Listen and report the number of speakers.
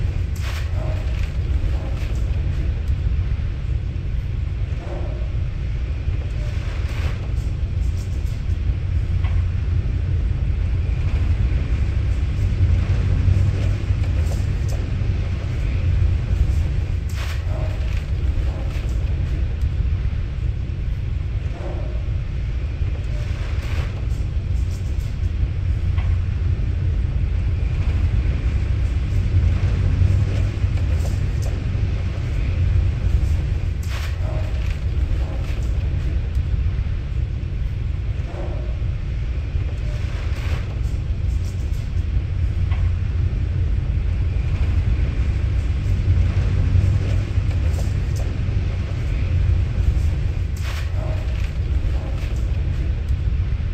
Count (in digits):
0